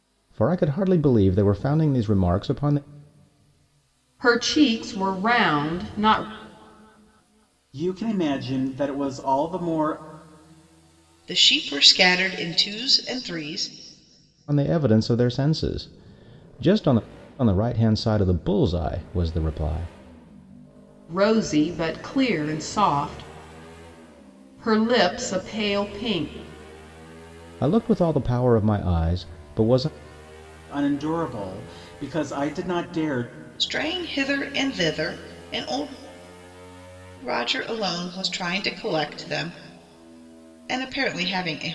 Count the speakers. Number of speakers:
4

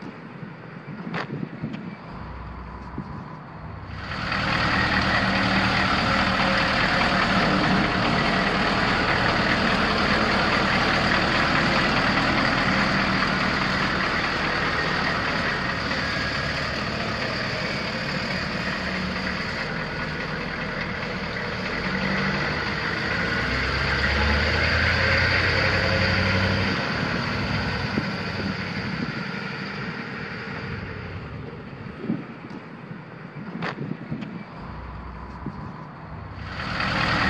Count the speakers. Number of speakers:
0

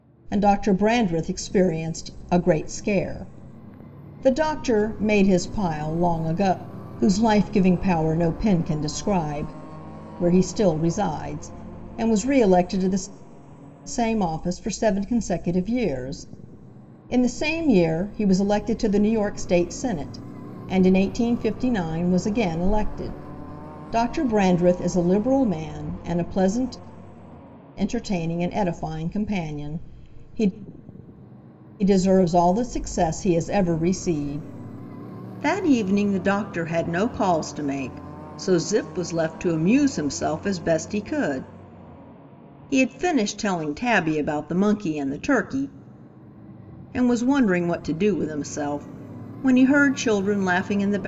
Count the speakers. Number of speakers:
1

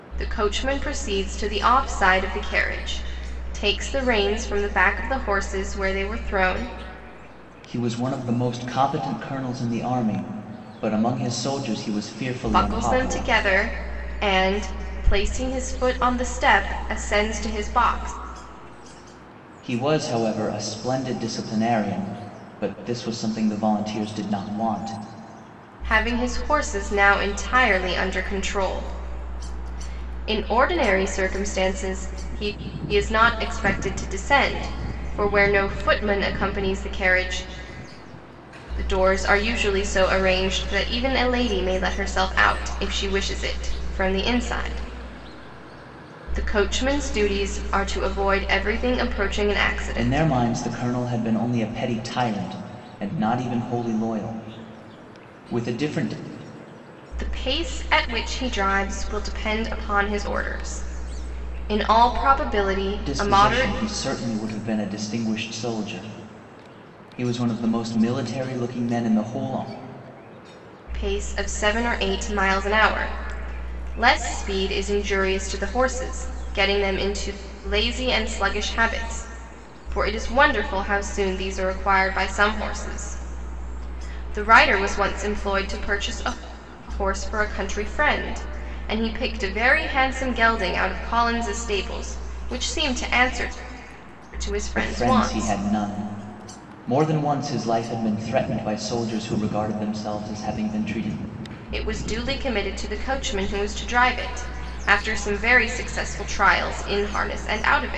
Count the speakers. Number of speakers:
2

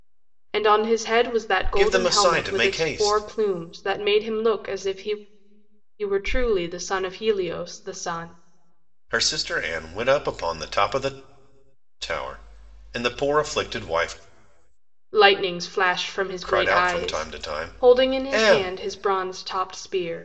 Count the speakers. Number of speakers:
2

